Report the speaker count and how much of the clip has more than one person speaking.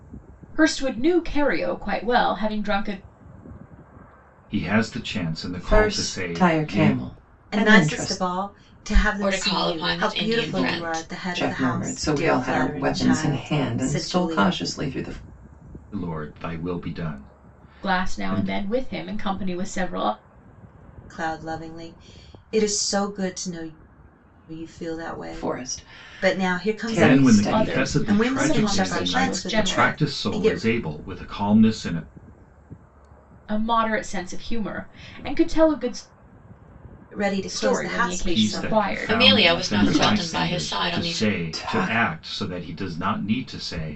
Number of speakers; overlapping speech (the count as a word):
five, about 42%